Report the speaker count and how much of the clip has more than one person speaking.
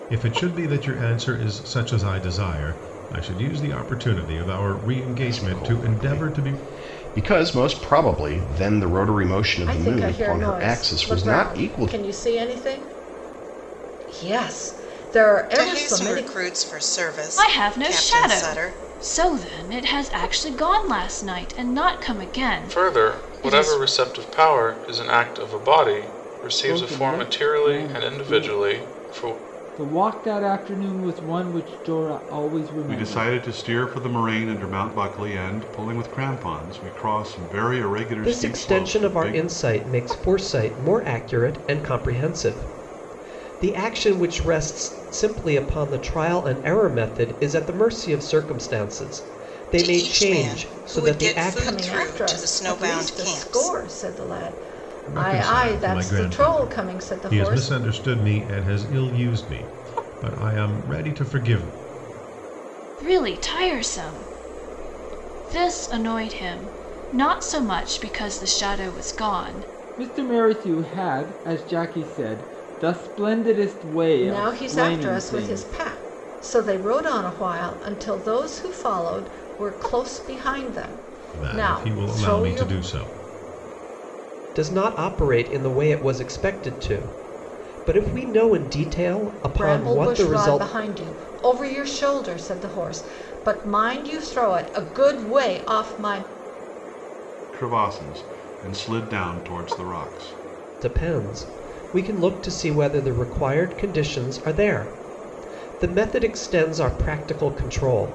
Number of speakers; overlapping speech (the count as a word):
nine, about 21%